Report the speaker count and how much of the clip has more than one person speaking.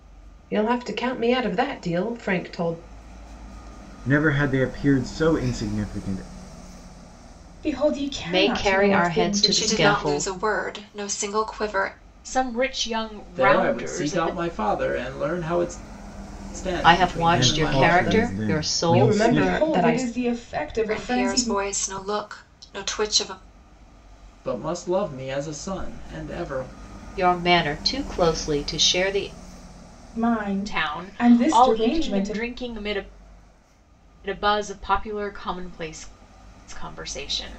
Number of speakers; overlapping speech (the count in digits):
7, about 24%